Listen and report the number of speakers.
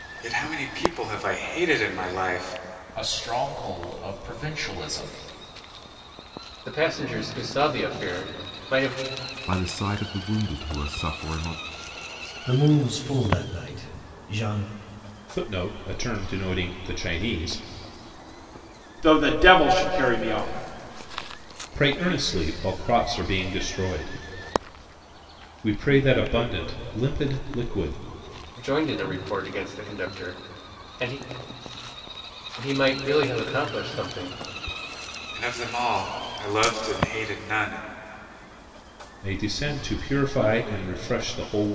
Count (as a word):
seven